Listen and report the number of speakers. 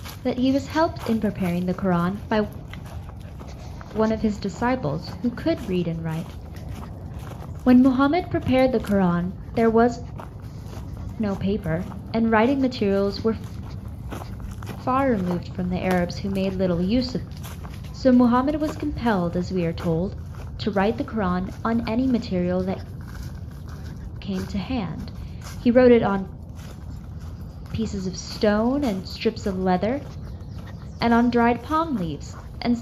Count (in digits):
1